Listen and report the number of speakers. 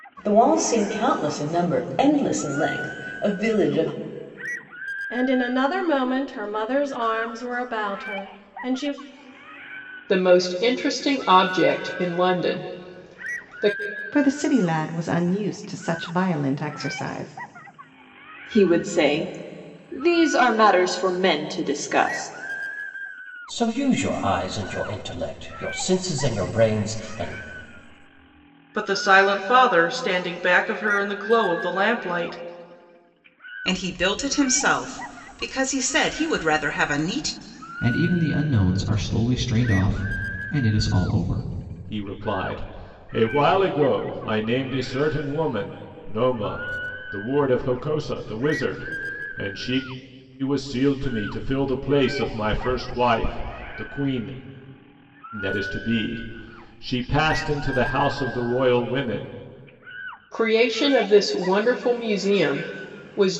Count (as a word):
ten